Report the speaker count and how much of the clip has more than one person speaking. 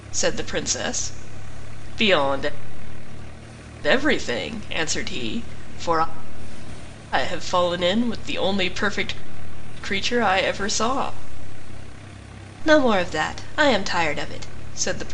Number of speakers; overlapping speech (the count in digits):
1, no overlap